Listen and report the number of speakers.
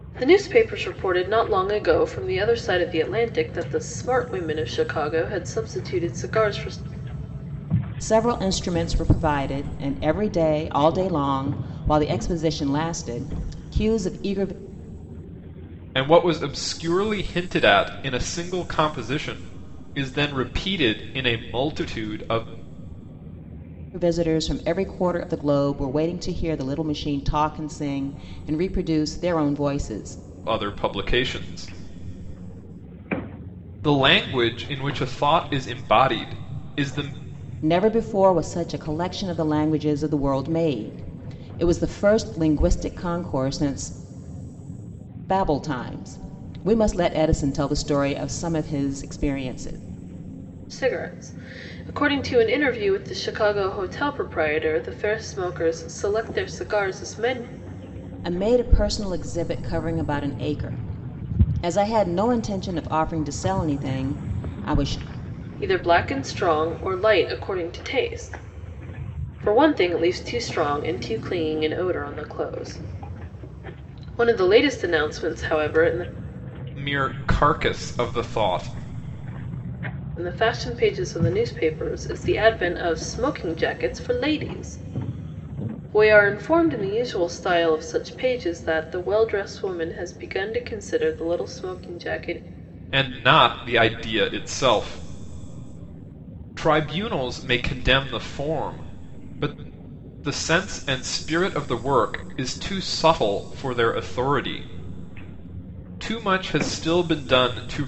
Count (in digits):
3